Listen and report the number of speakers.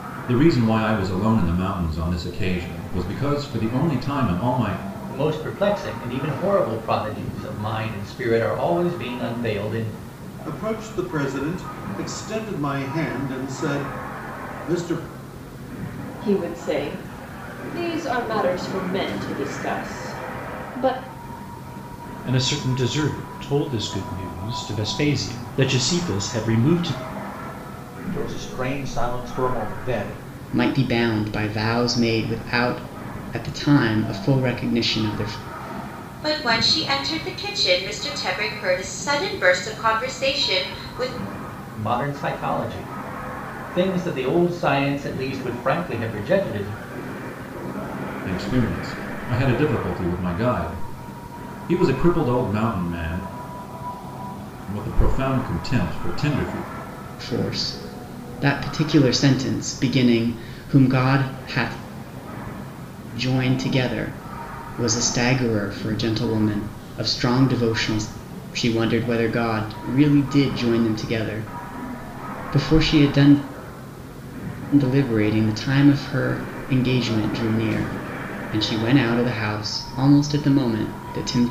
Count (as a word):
eight